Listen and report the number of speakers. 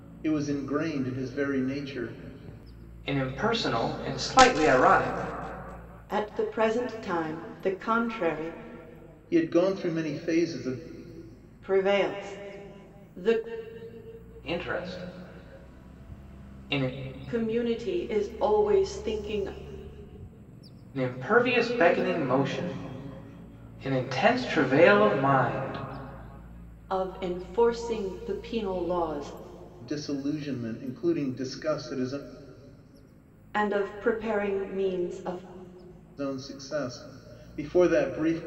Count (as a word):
three